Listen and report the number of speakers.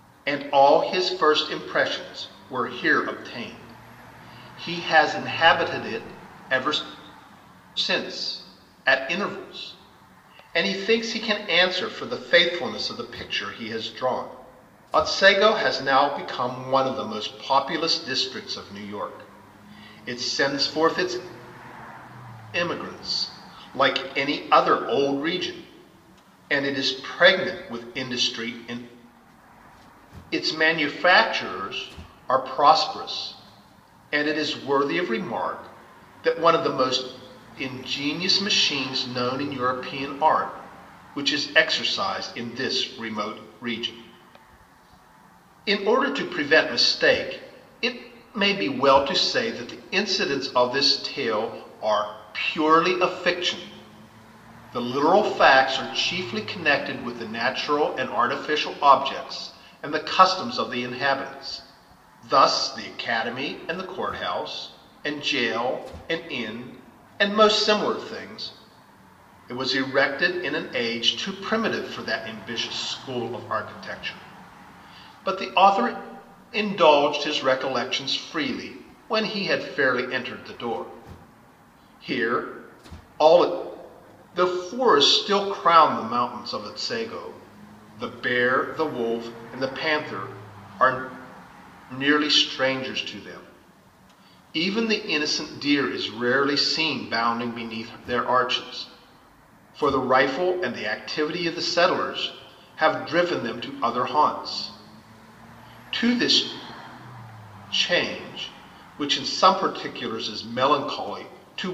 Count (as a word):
one